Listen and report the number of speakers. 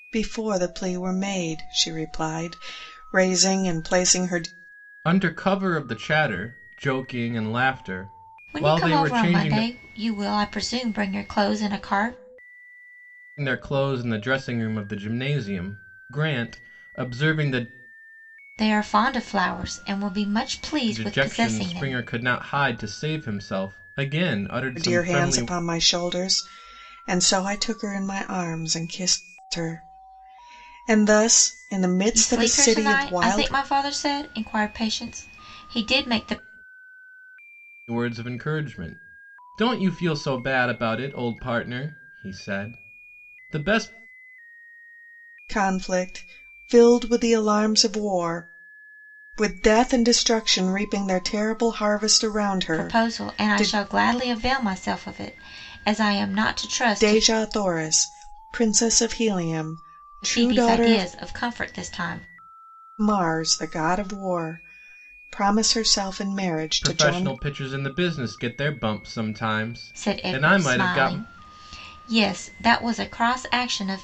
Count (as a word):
three